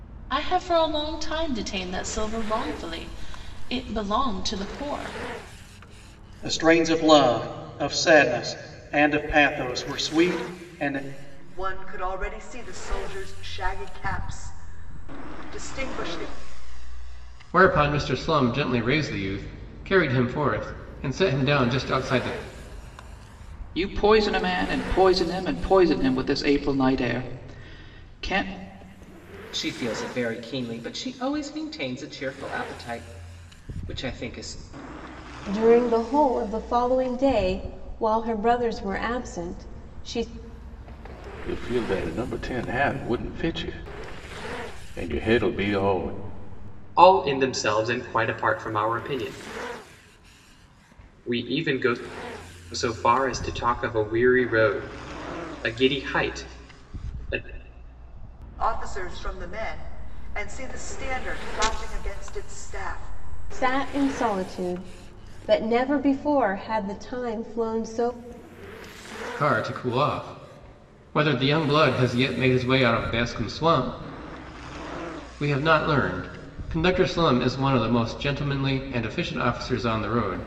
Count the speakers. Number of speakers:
9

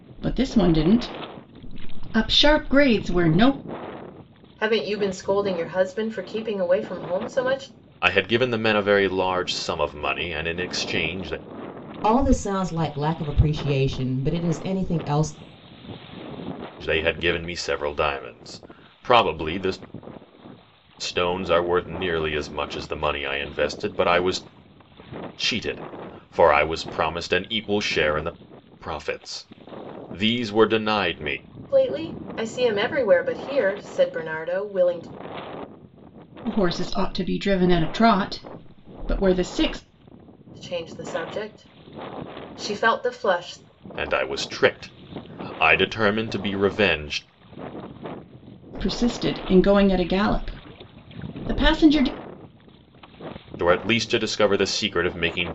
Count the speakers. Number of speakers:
4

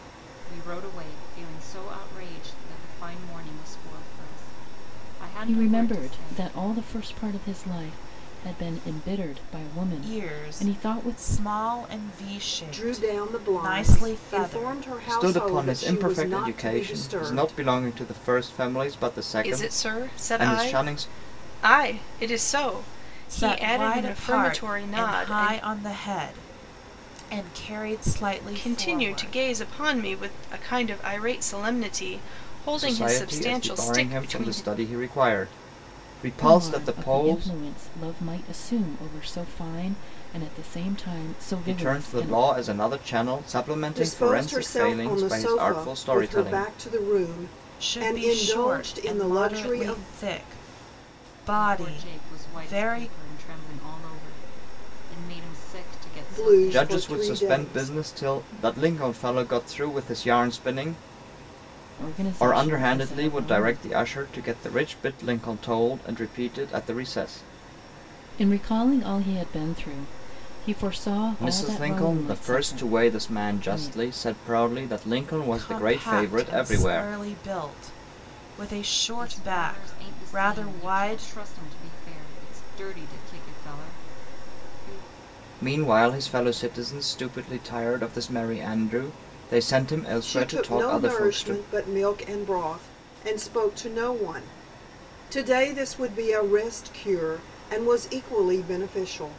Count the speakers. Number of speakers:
6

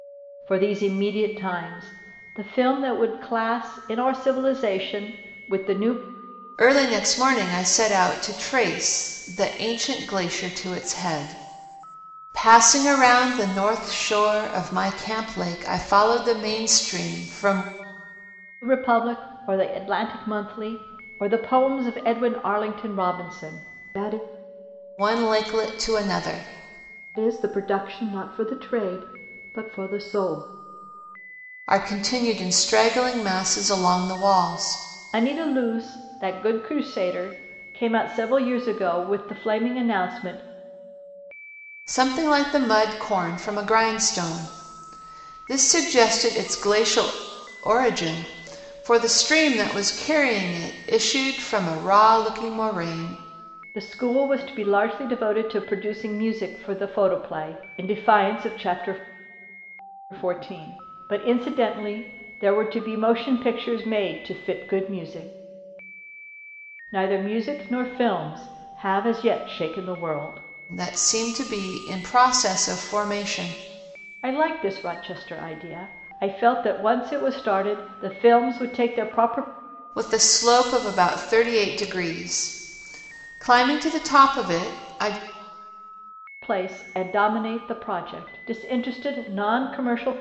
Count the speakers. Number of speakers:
2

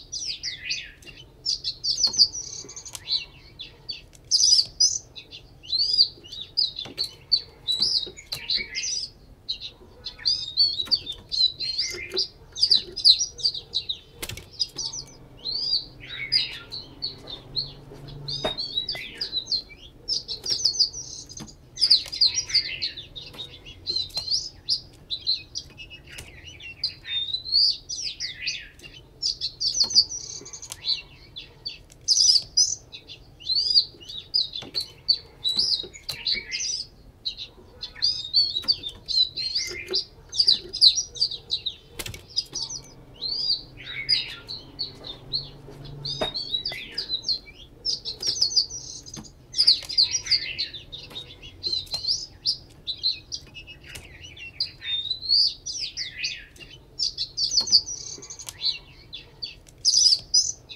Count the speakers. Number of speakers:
0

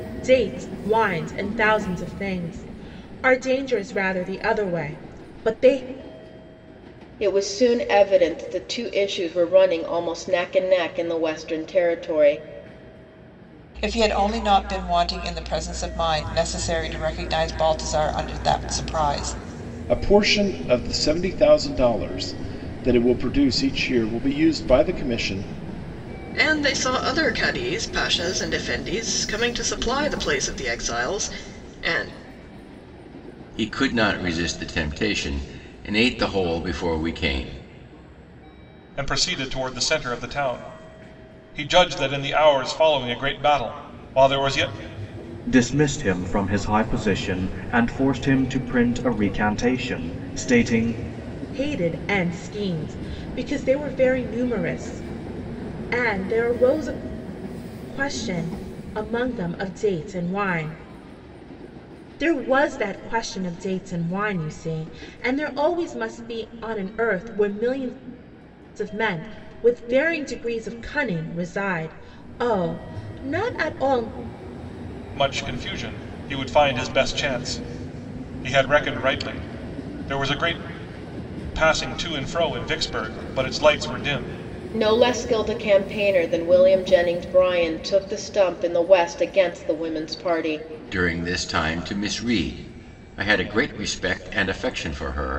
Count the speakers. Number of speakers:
8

